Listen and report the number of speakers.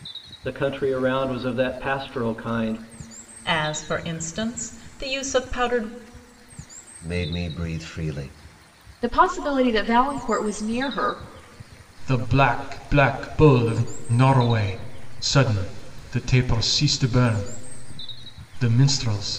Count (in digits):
5